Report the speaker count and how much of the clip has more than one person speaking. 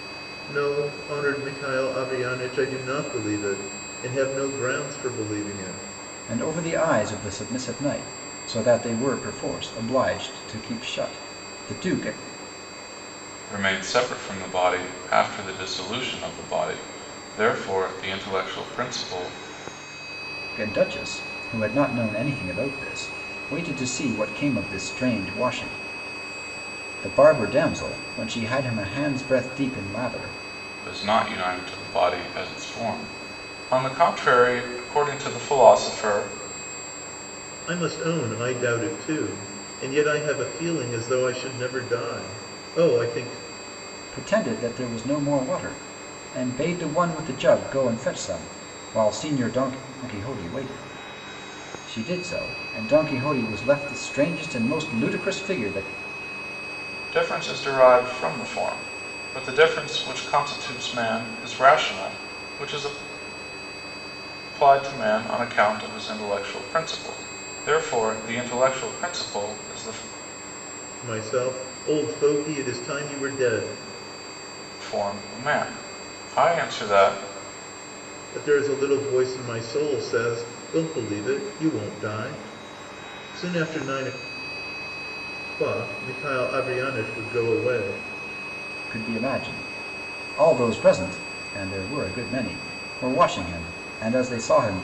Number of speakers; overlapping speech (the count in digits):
3, no overlap